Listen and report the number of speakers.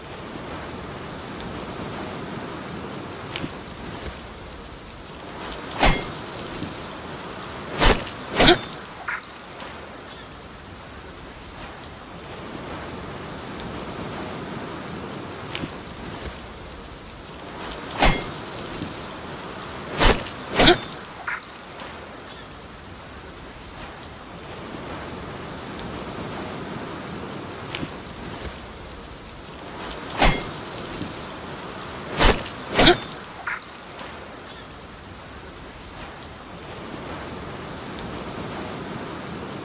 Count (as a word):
zero